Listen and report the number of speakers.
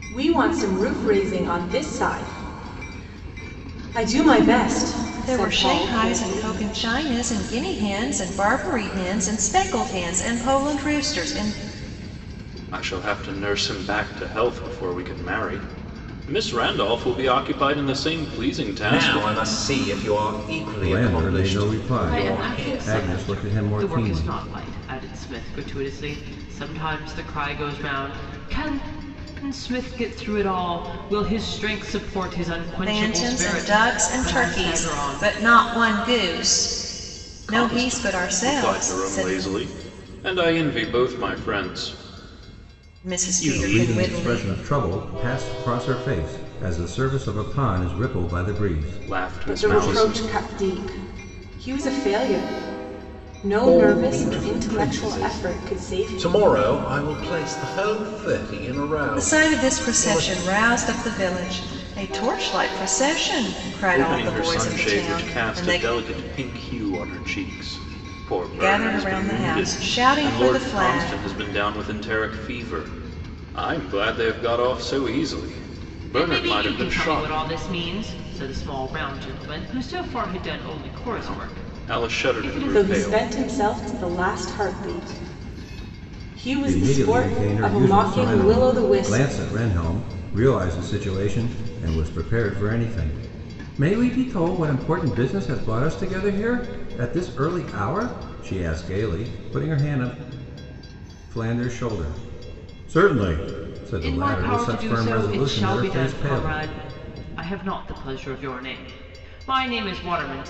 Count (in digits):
6